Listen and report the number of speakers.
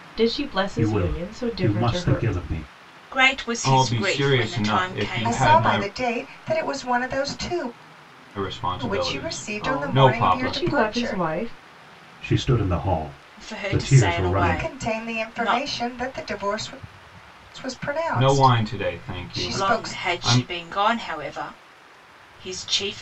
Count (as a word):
five